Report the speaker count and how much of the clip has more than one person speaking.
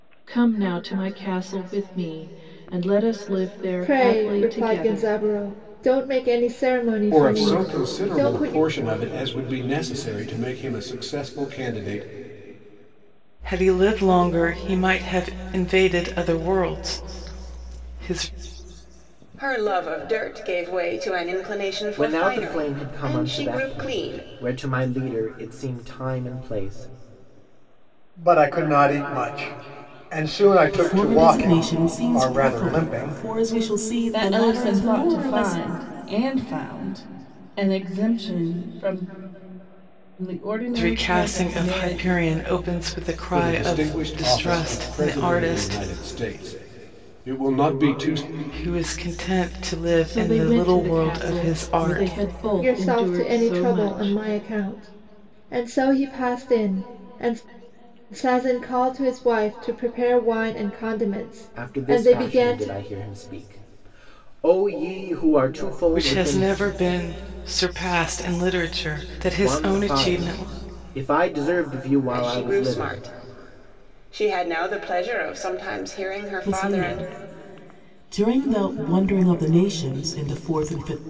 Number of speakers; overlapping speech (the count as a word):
nine, about 27%